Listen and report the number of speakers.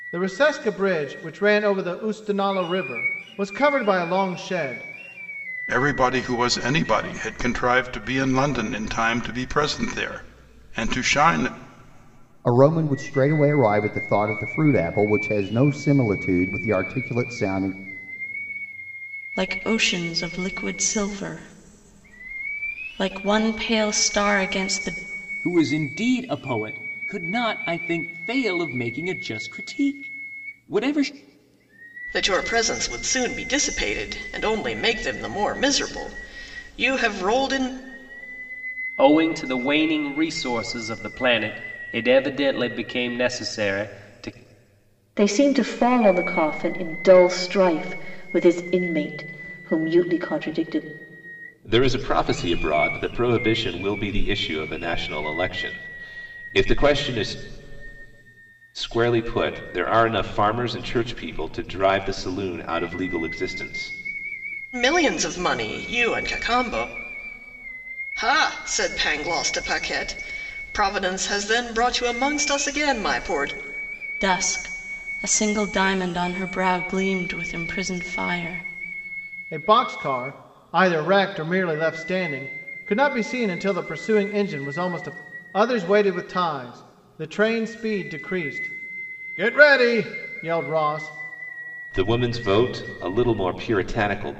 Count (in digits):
9